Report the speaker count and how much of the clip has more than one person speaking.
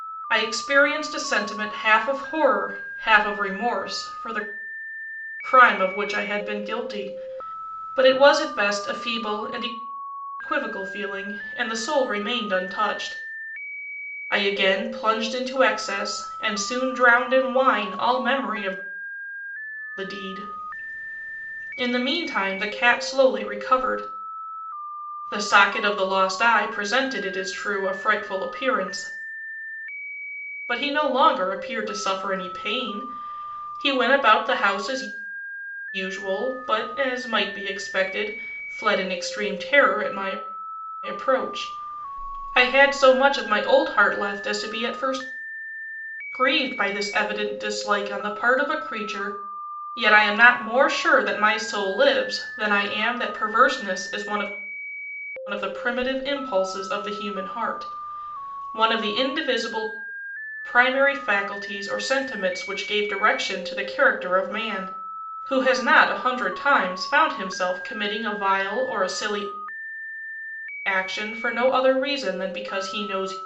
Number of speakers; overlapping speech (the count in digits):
1, no overlap